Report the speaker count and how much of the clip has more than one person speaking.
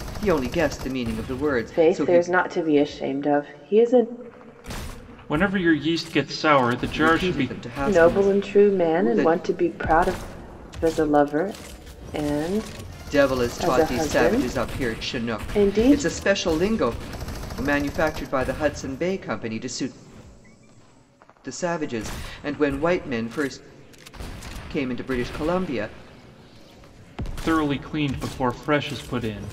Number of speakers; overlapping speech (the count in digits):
3, about 17%